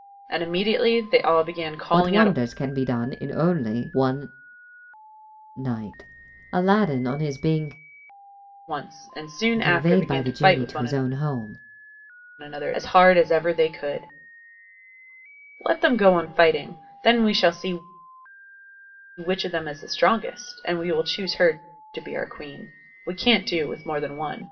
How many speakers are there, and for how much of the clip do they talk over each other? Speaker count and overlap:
2, about 8%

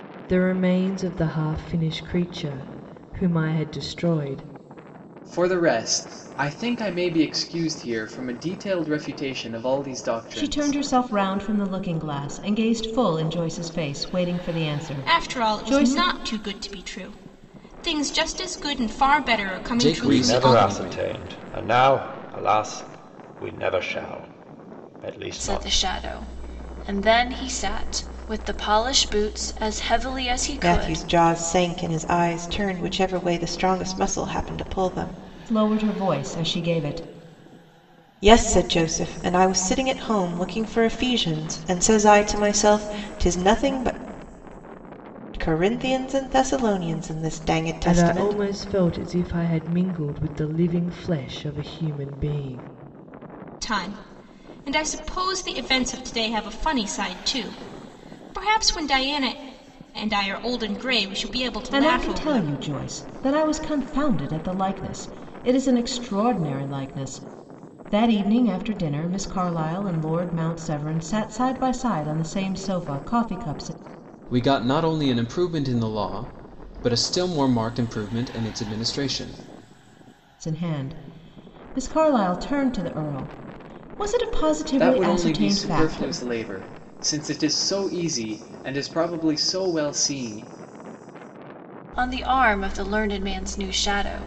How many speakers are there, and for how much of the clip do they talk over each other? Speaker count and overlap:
8, about 7%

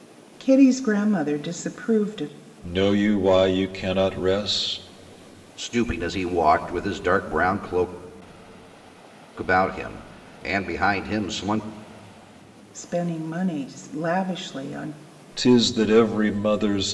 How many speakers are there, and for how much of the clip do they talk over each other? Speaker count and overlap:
3, no overlap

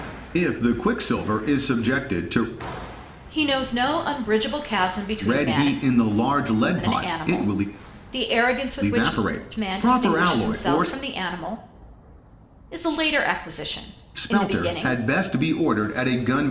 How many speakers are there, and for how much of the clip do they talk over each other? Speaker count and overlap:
2, about 24%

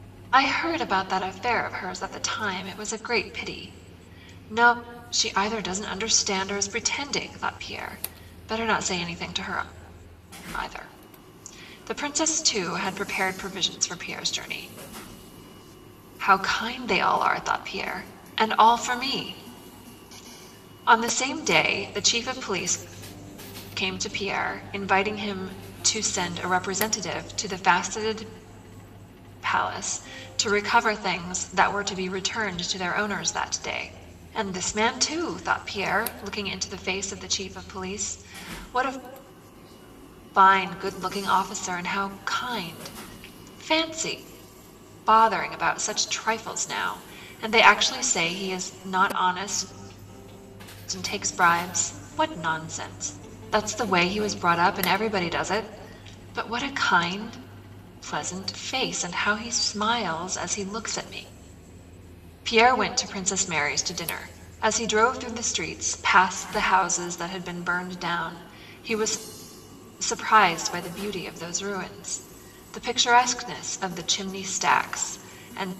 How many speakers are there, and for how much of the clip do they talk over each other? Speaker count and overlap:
1, no overlap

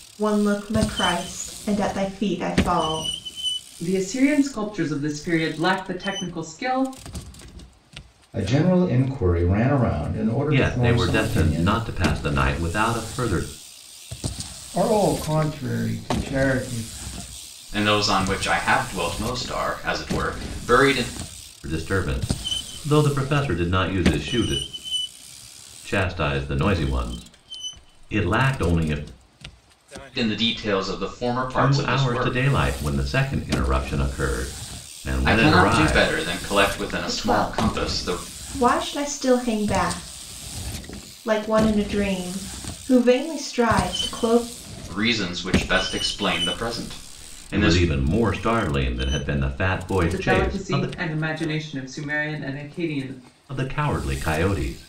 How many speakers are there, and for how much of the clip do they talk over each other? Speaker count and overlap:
6, about 10%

